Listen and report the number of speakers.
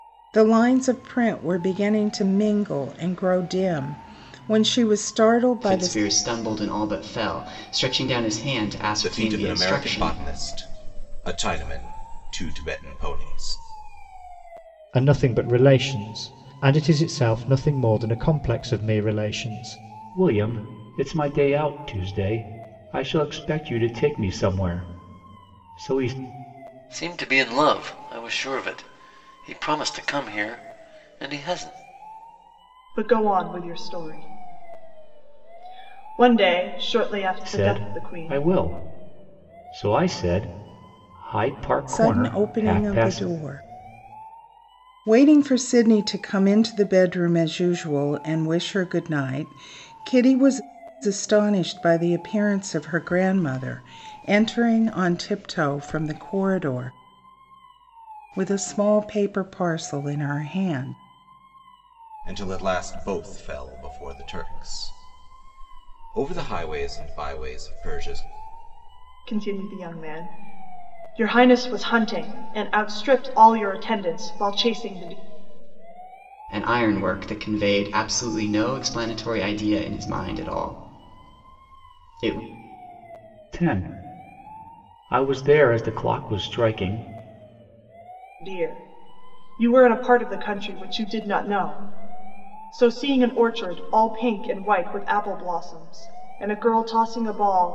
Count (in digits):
7